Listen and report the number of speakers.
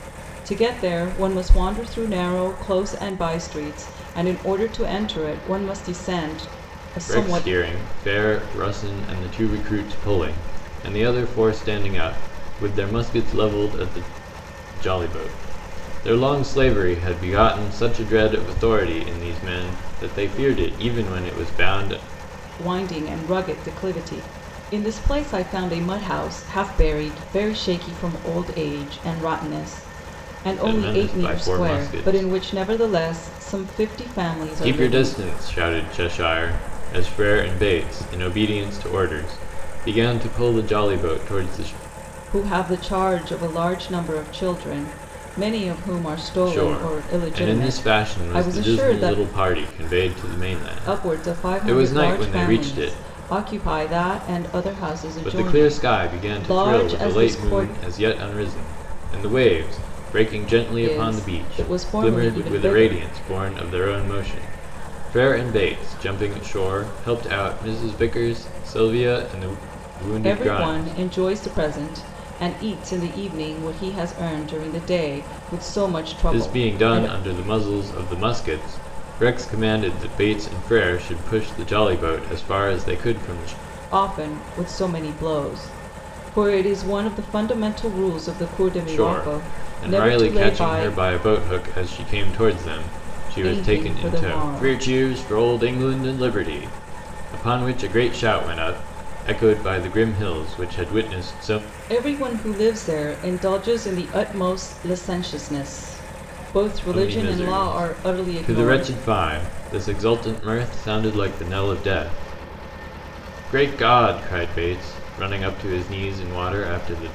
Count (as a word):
two